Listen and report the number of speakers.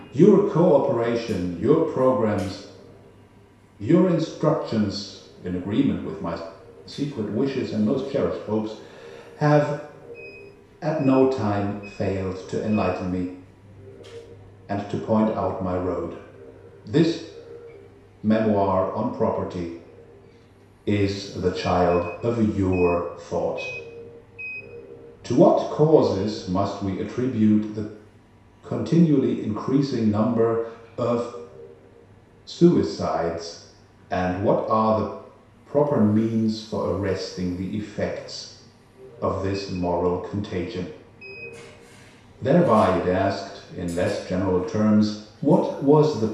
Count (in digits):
1